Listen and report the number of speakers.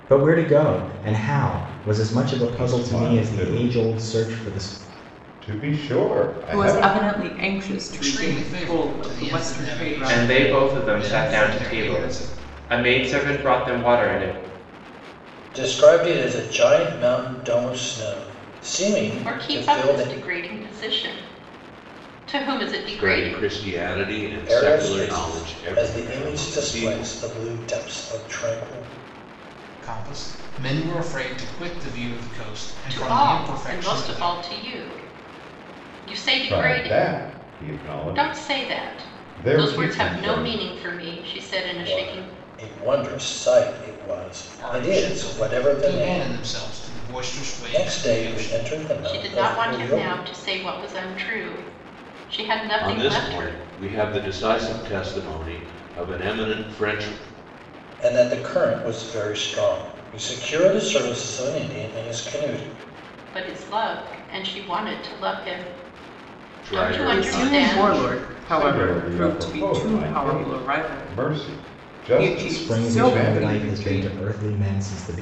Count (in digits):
8